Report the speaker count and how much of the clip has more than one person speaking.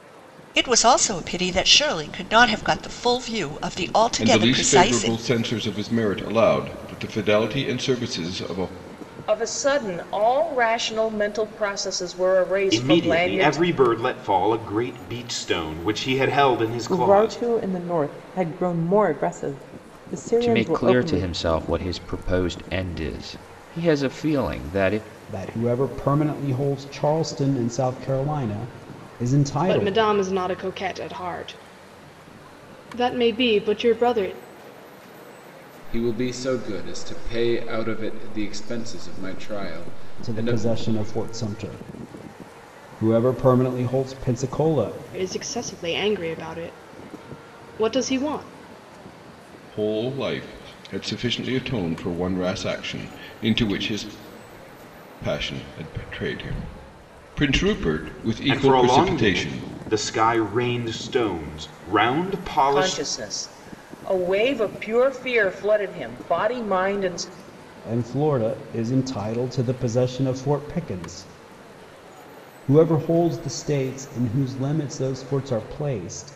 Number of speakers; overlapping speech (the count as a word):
nine, about 8%